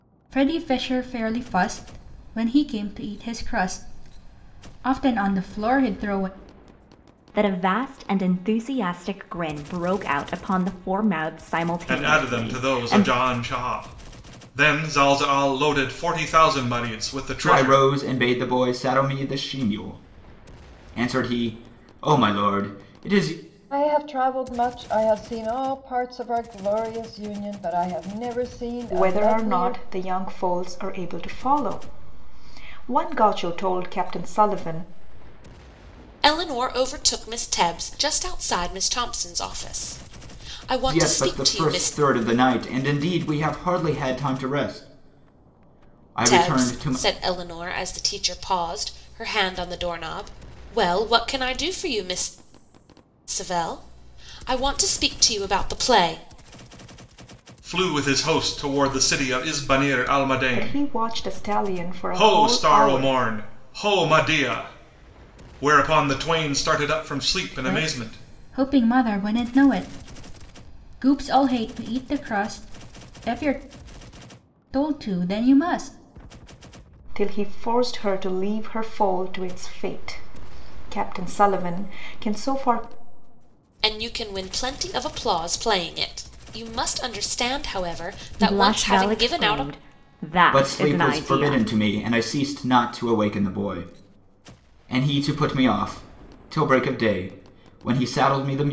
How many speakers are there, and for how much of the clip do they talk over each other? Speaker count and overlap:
7, about 9%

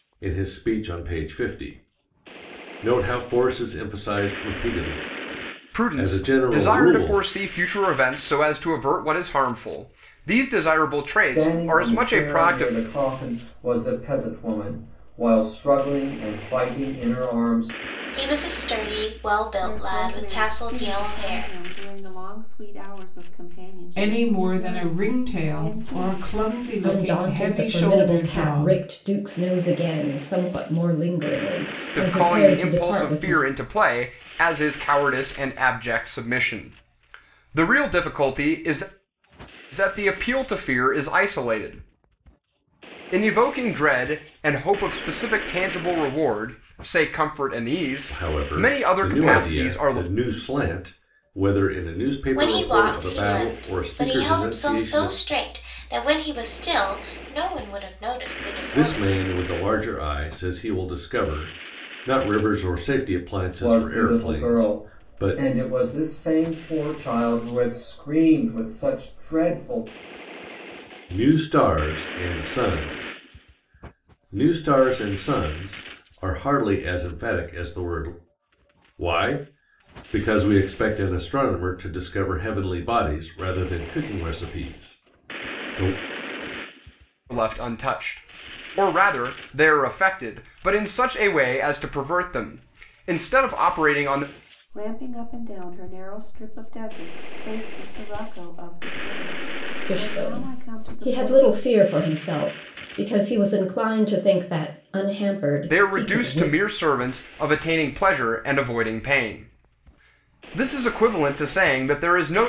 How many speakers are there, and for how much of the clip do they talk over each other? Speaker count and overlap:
7, about 19%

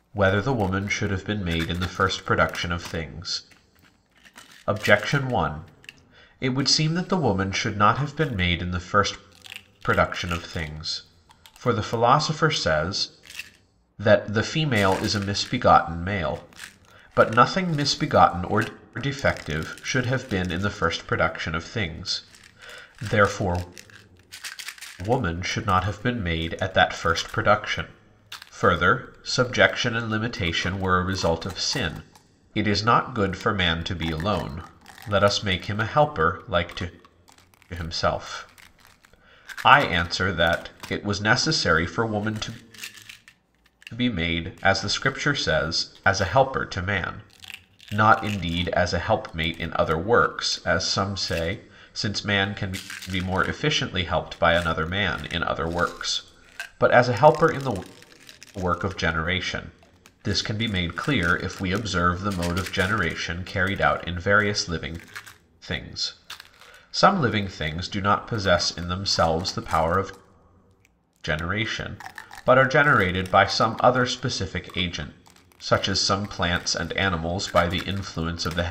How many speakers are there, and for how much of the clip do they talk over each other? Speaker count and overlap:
1, no overlap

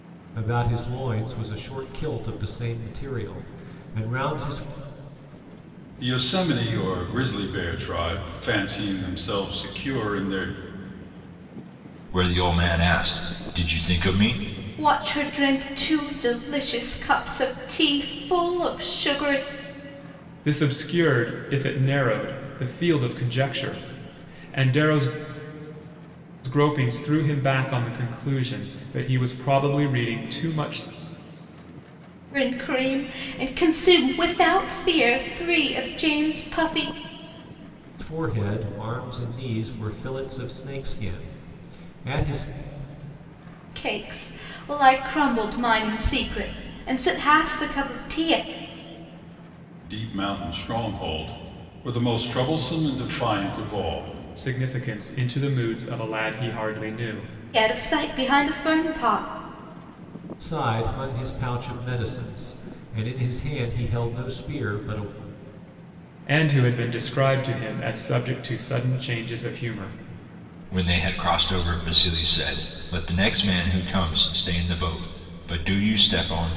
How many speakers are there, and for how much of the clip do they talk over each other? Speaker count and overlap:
5, no overlap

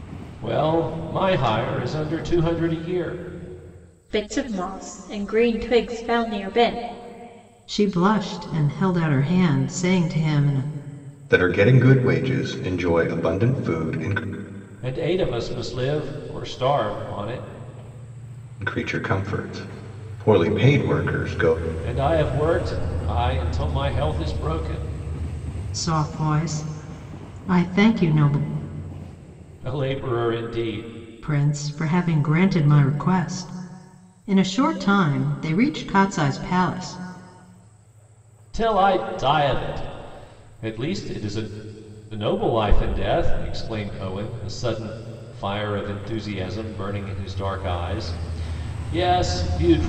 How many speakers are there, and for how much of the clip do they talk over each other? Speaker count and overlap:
4, no overlap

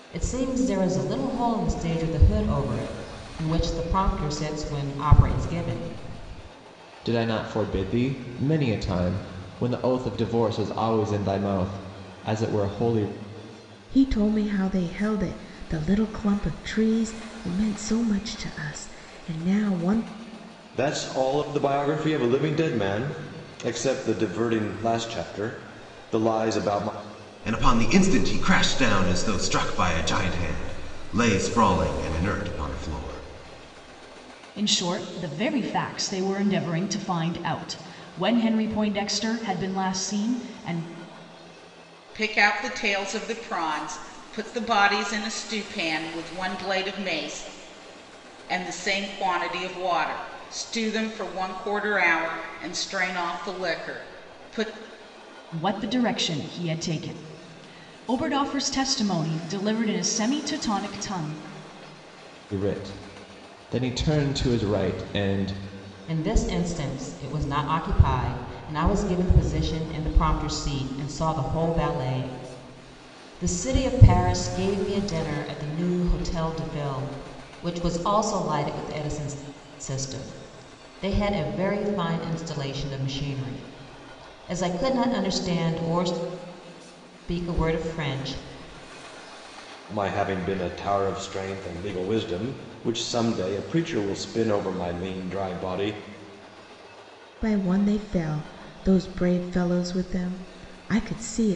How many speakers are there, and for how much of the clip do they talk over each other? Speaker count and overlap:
7, no overlap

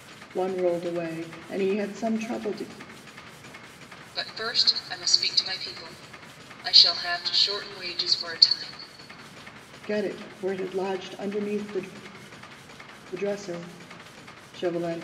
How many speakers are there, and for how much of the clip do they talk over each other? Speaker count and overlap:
2, no overlap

